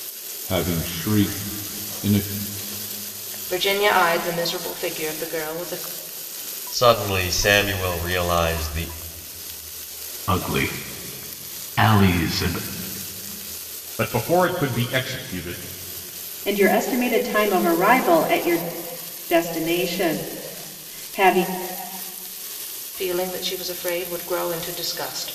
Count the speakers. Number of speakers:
6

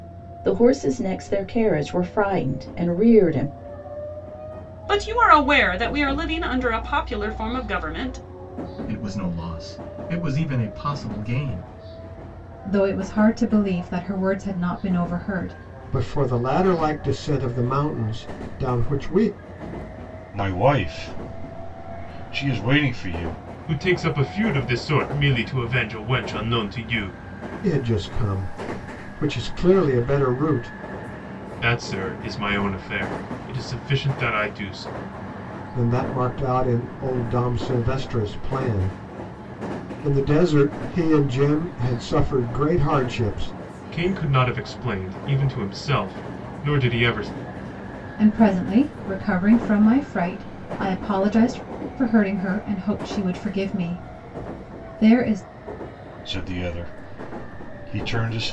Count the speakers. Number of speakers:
7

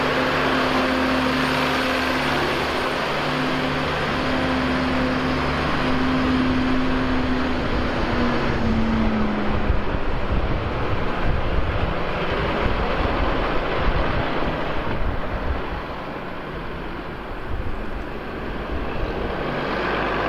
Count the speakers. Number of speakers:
0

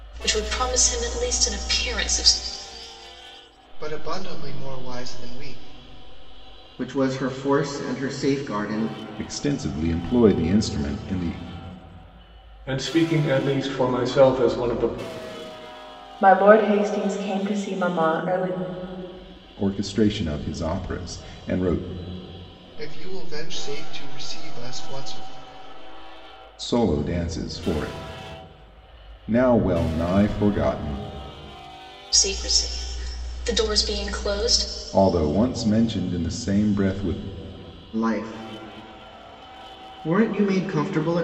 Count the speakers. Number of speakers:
6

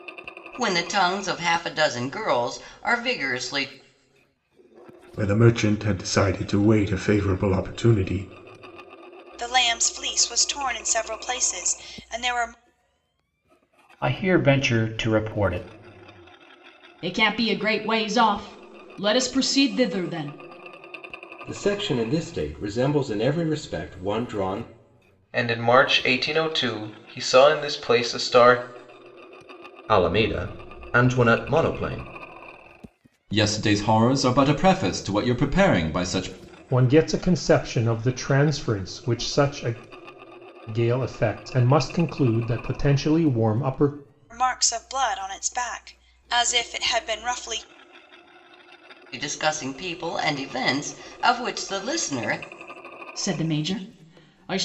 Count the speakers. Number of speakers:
10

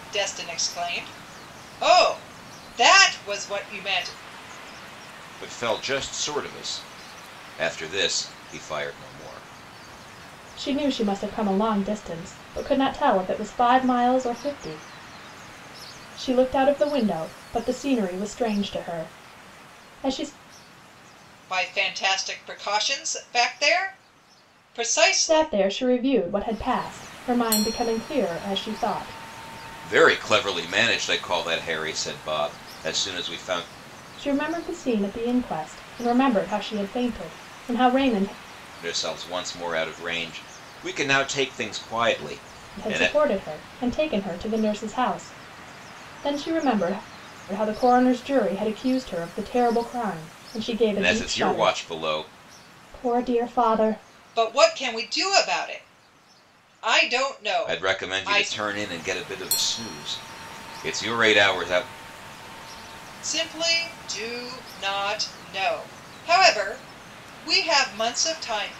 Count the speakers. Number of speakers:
3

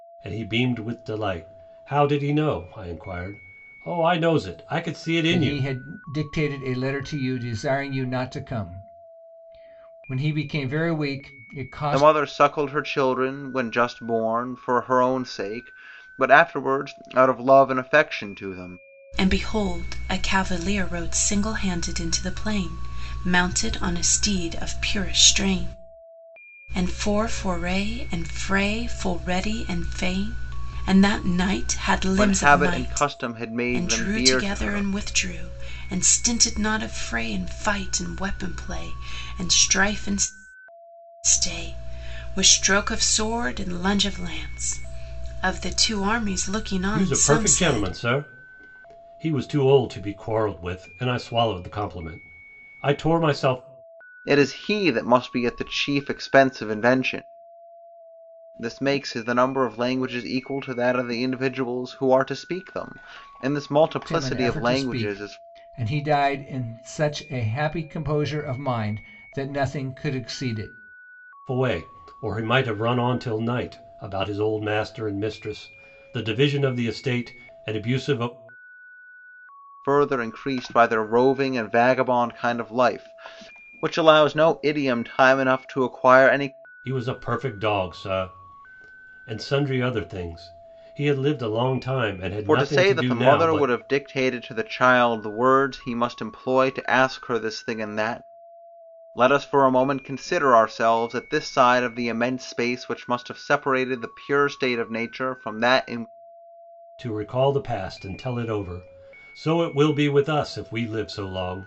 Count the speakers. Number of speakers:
4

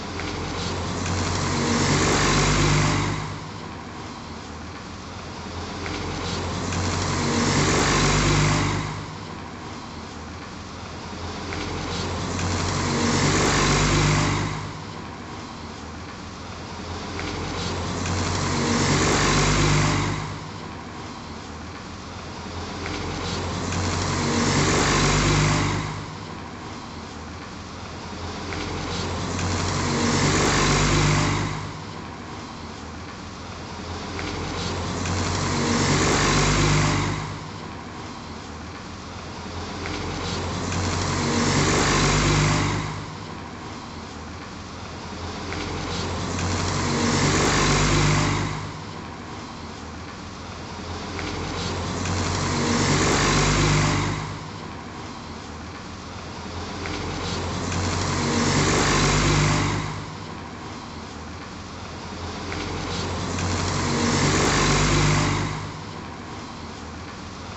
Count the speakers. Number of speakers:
0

